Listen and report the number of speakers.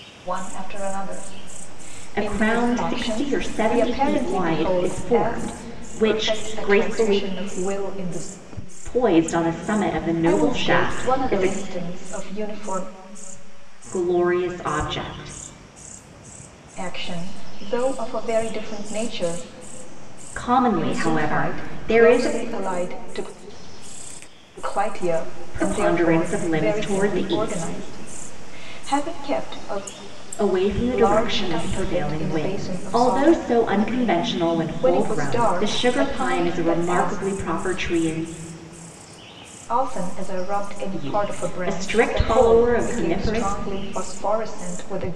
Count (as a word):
two